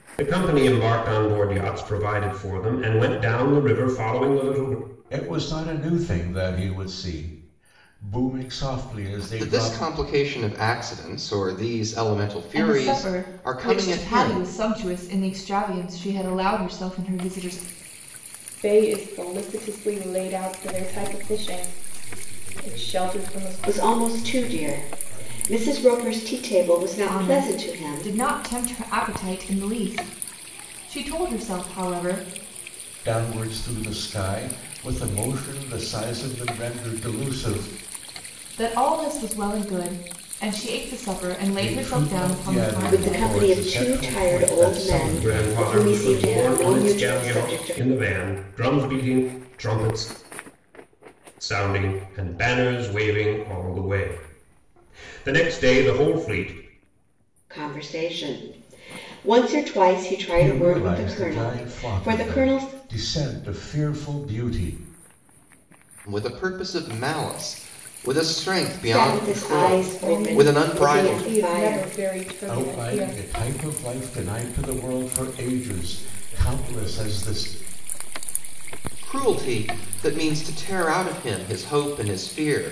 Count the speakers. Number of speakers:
7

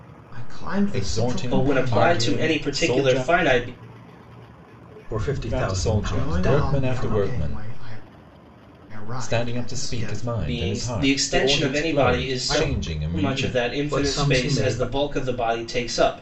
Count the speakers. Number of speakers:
4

